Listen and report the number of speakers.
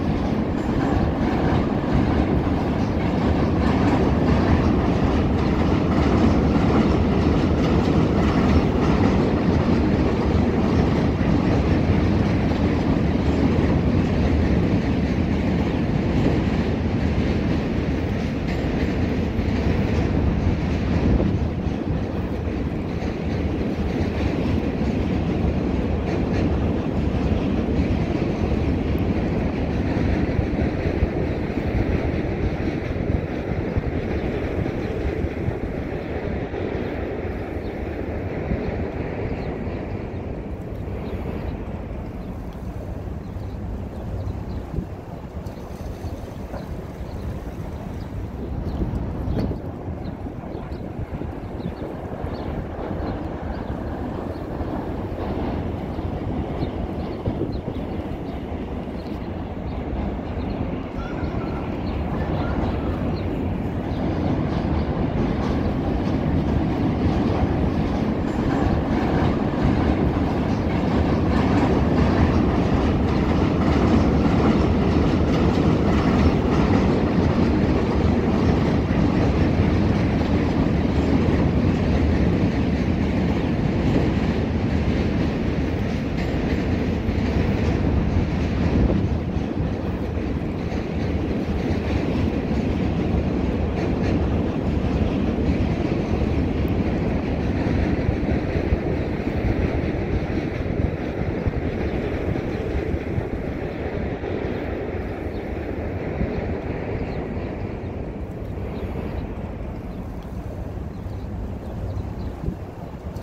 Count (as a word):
zero